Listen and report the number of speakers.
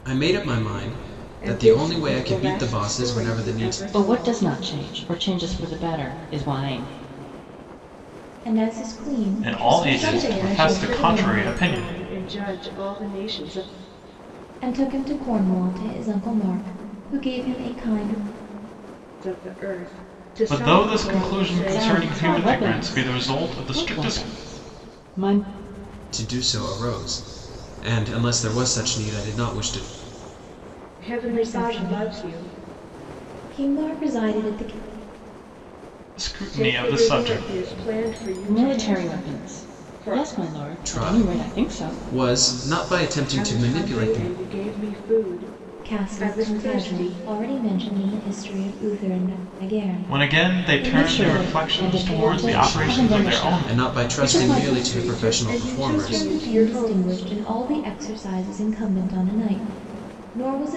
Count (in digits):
5